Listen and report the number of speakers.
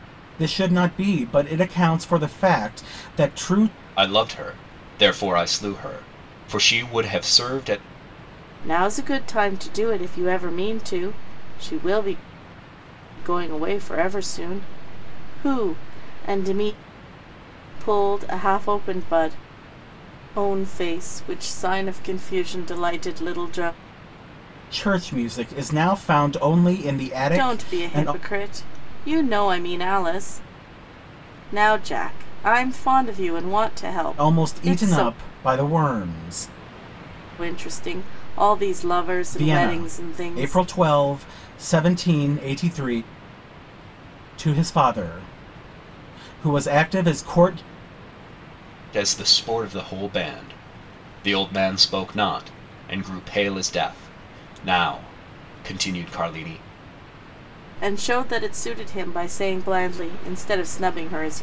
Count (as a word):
three